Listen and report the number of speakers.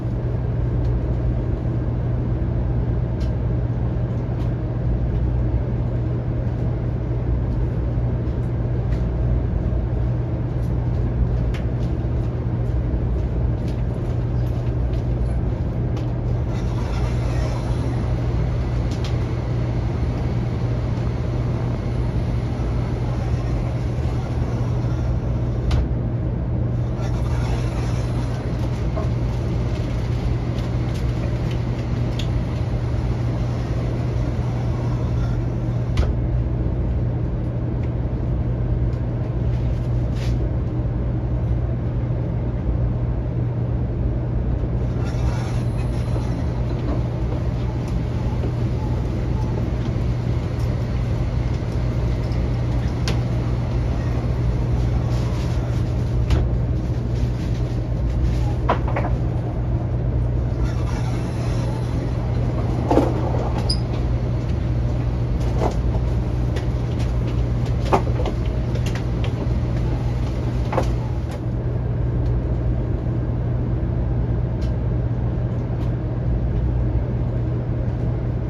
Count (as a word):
zero